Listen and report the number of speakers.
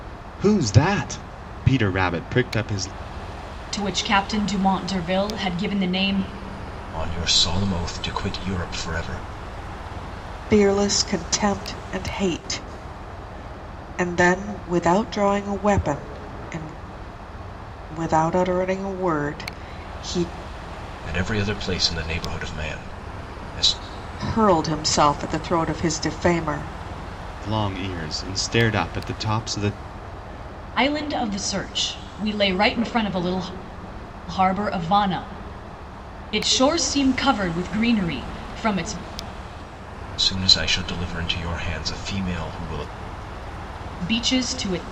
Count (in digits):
4